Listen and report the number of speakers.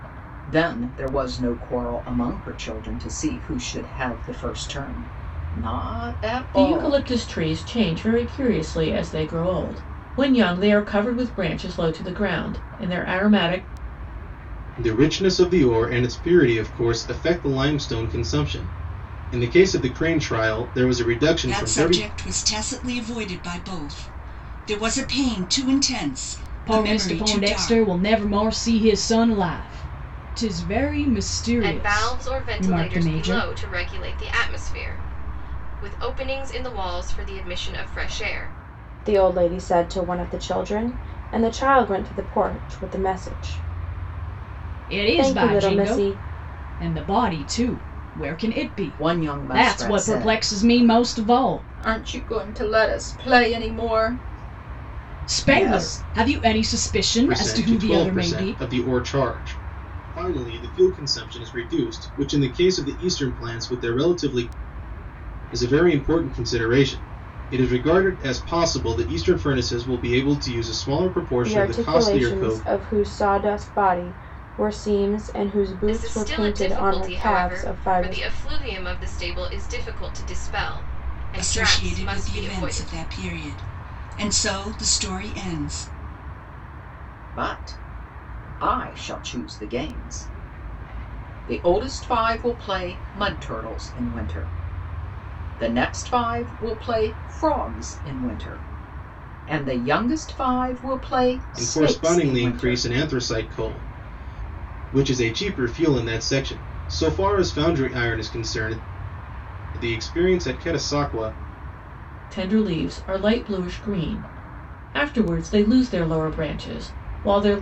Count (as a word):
seven